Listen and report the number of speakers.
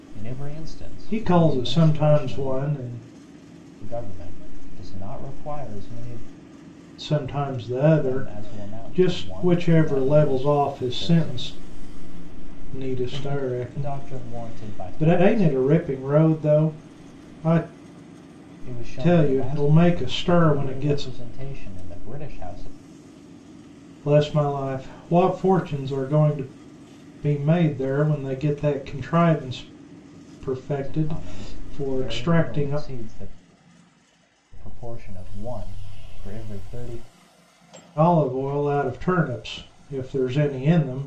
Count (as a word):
two